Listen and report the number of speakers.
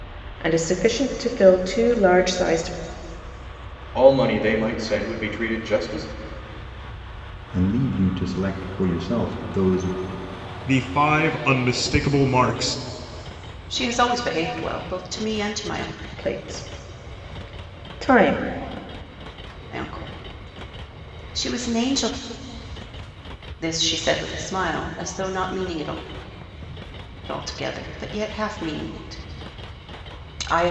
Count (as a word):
five